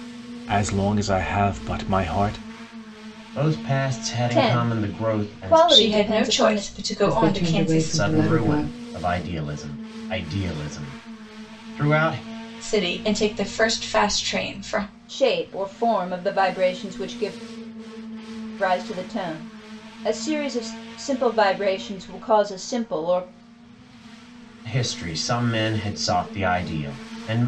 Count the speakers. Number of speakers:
five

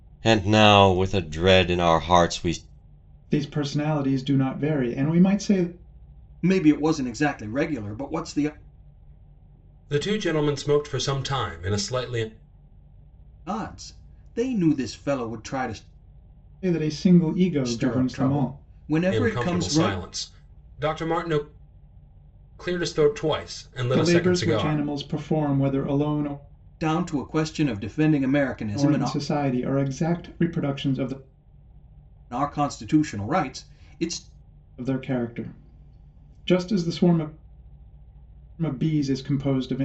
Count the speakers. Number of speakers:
four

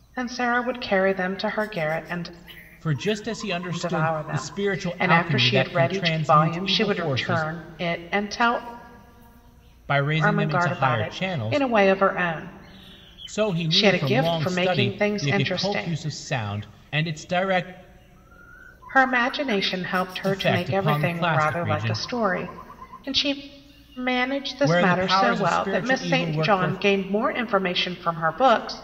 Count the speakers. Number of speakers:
two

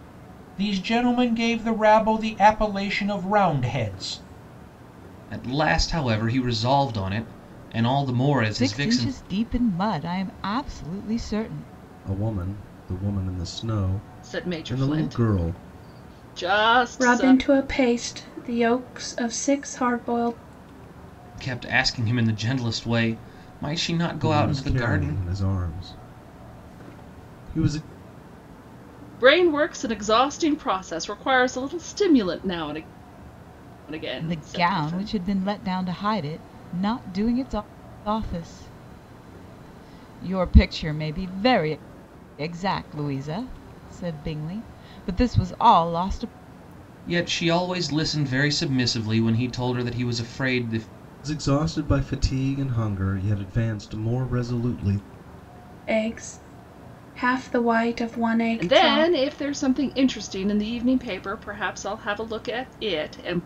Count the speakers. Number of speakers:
six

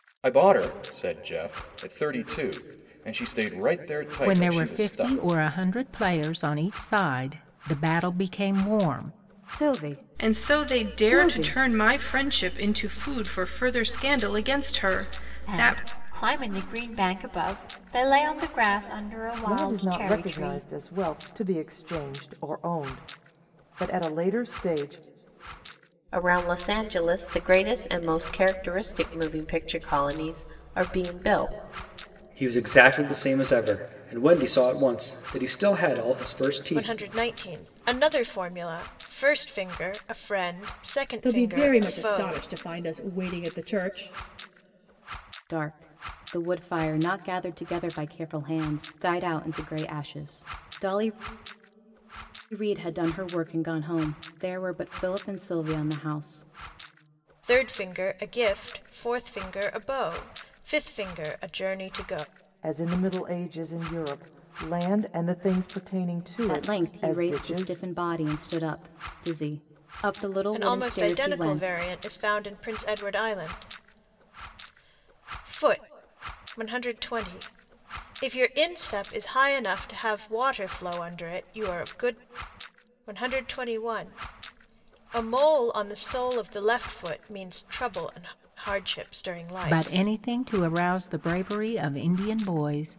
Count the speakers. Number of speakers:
ten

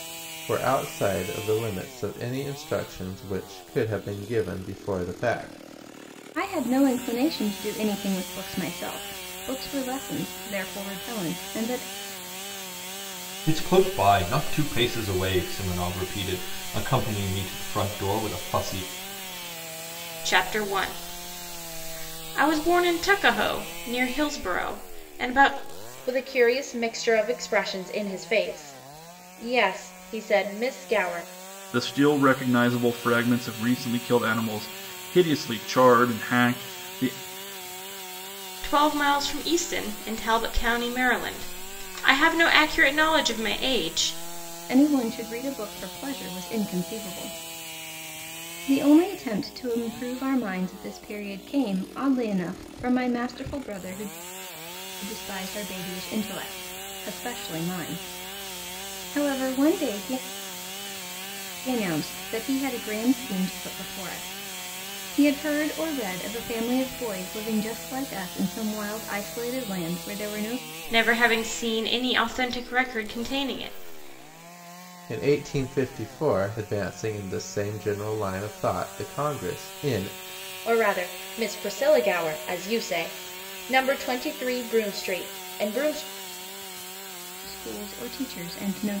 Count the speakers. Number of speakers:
six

